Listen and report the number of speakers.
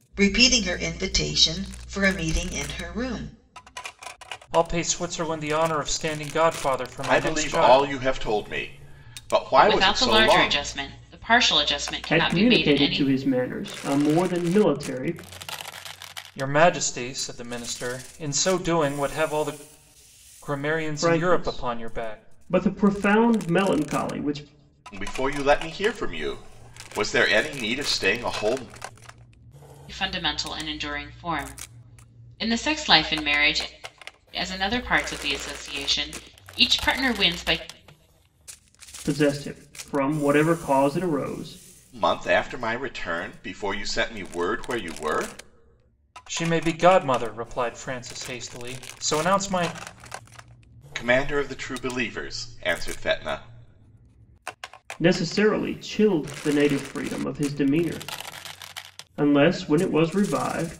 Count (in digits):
5